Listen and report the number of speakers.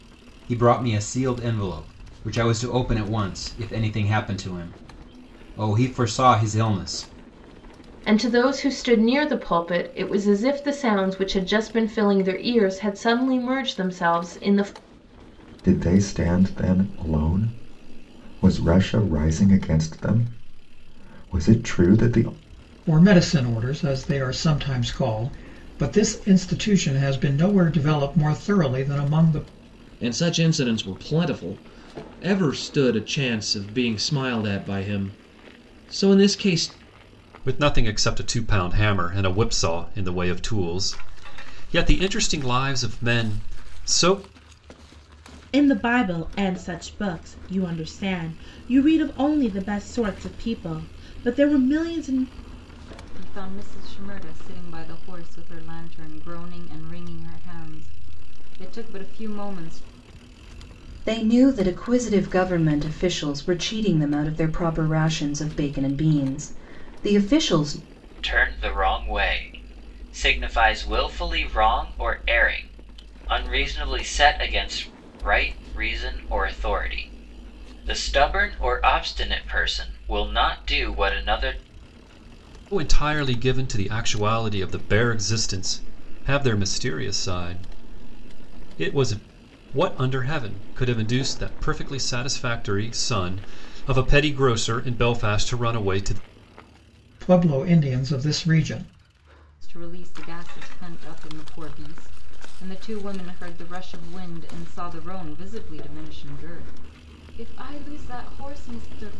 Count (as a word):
ten